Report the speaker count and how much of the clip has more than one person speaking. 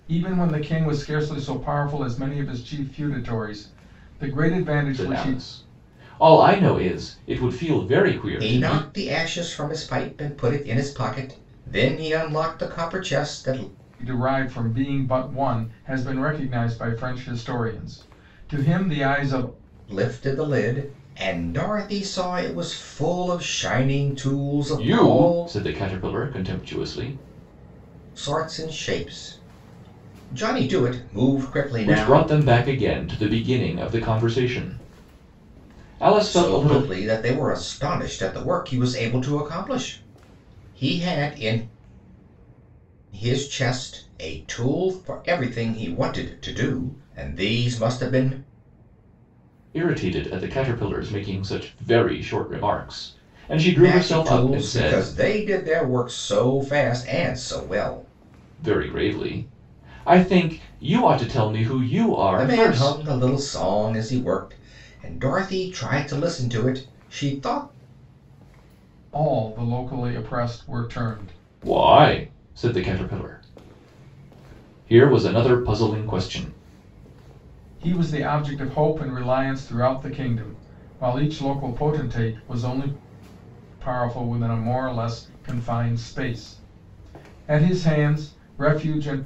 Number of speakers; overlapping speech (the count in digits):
3, about 5%